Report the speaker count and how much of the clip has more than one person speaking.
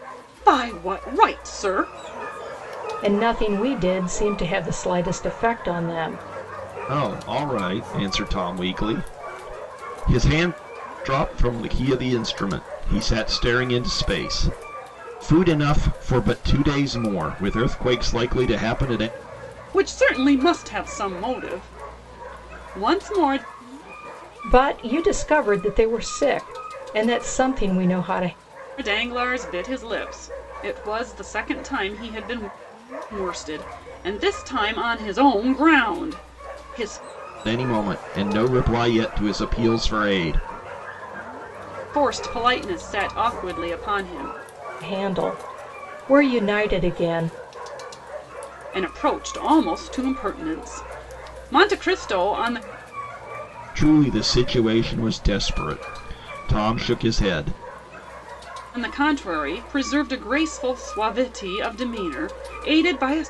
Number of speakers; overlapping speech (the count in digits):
3, no overlap